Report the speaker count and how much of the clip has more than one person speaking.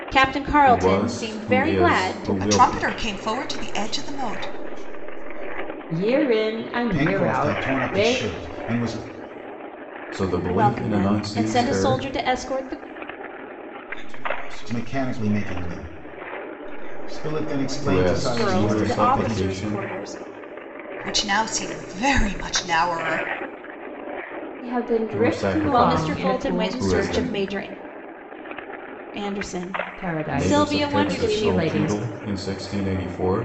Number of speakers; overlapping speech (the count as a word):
six, about 43%